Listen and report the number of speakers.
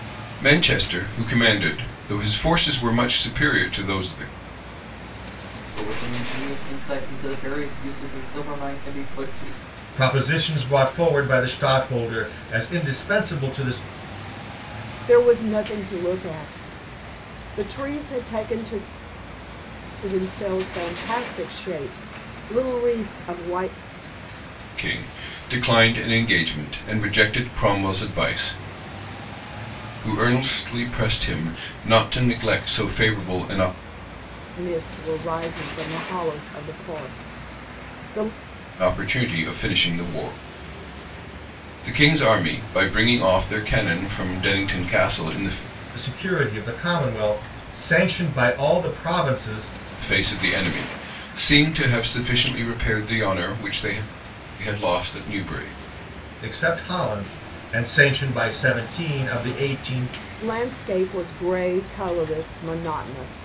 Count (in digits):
4